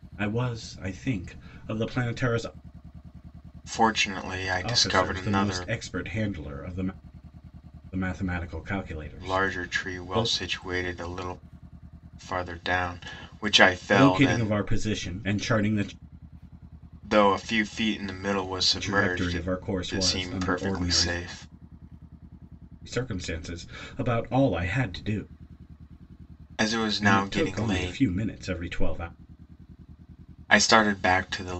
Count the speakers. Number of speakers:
two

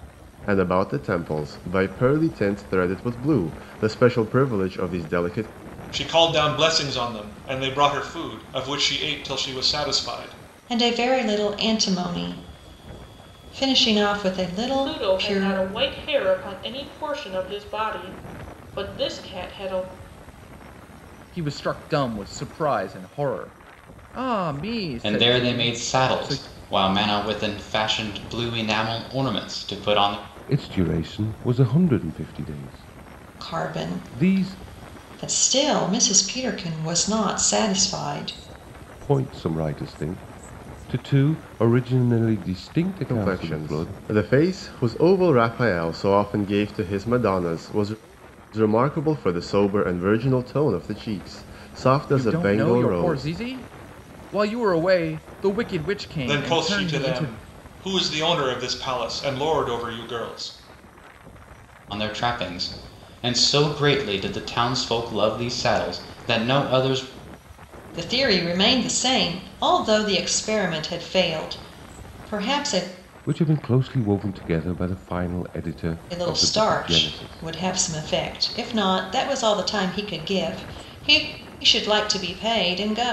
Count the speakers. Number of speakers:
seven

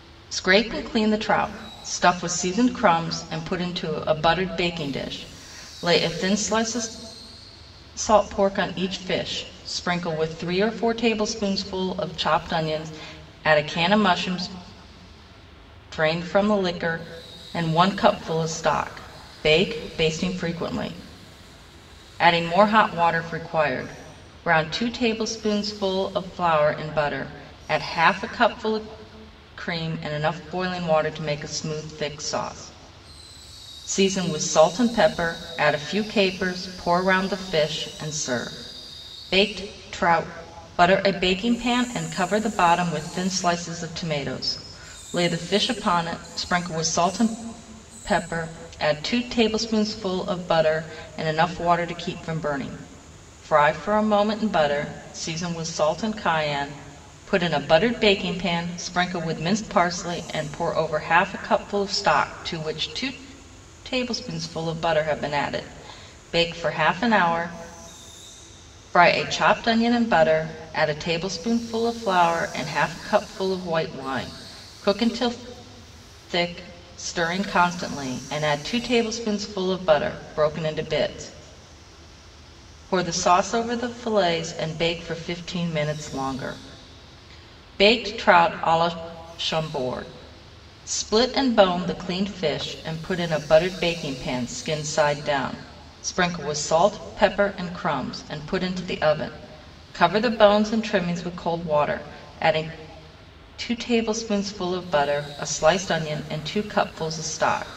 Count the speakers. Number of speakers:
one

